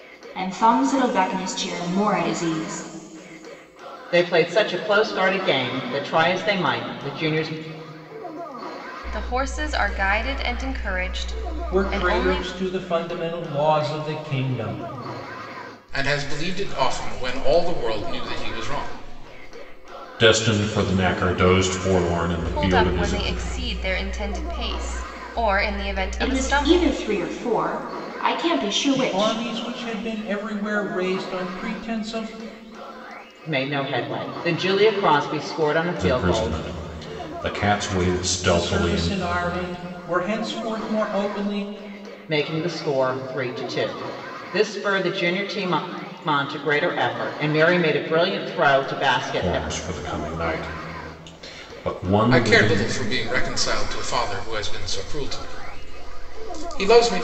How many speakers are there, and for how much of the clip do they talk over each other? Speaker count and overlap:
six, about 9%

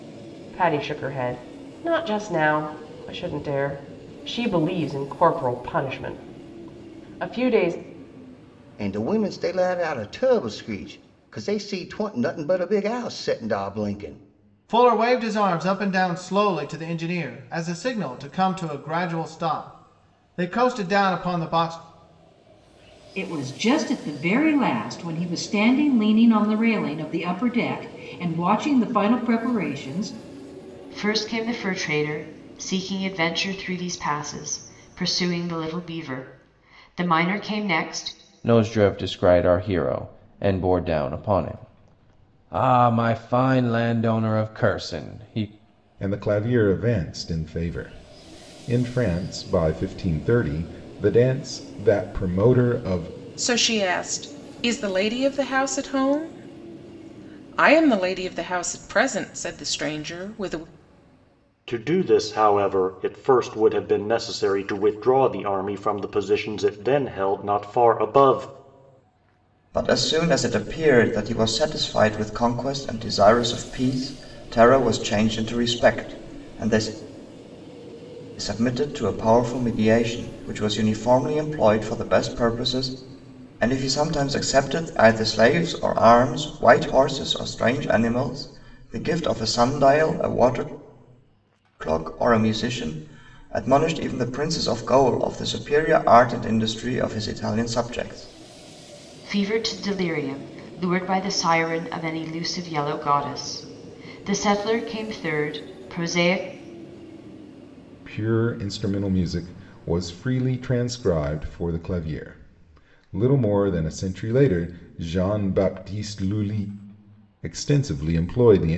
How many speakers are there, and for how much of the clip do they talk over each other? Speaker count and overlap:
ten, no overlap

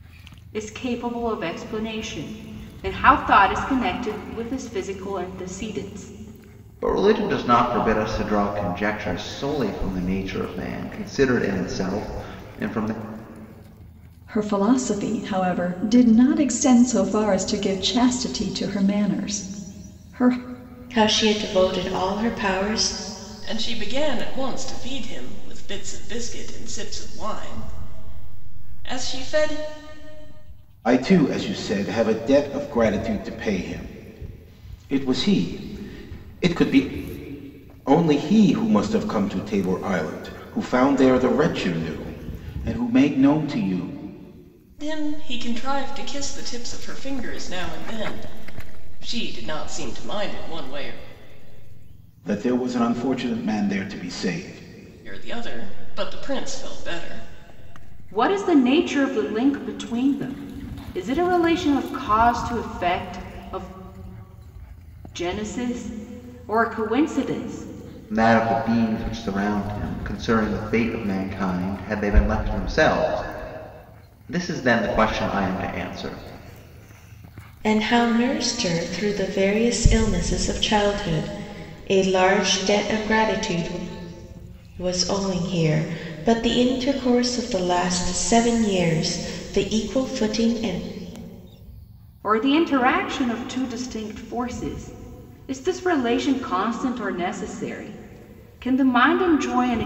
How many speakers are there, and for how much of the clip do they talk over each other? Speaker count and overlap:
six, no overlap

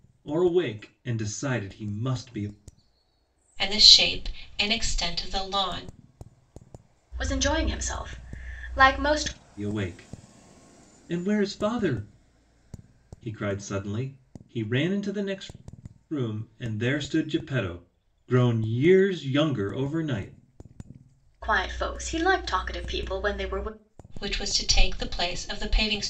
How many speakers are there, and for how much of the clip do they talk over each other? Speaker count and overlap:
three, no overlap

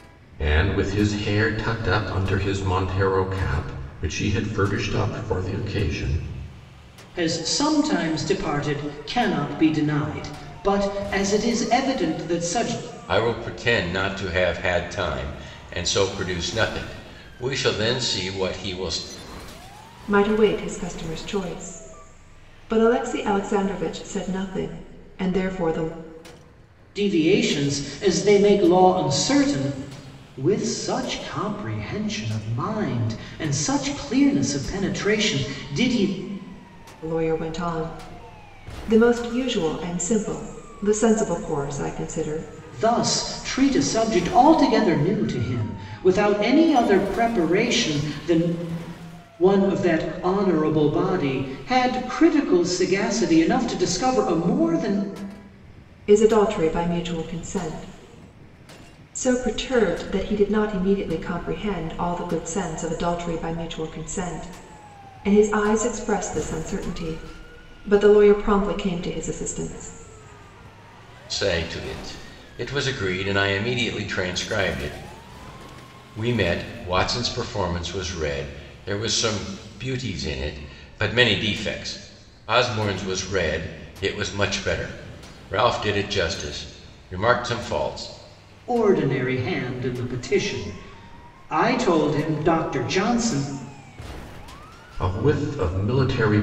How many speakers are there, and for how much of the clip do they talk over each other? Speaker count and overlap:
four, no overlap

